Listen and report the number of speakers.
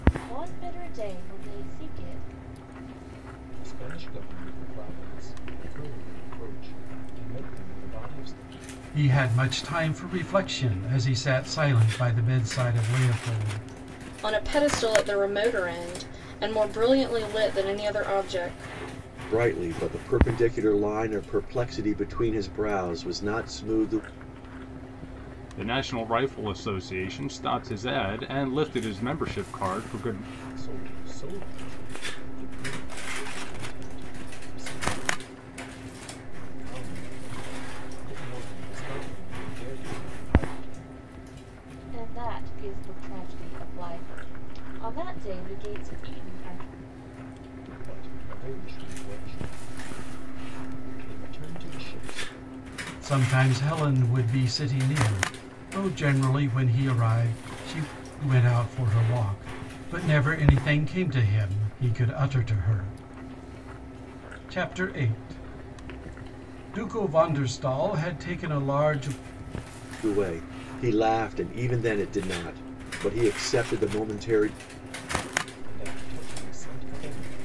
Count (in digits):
6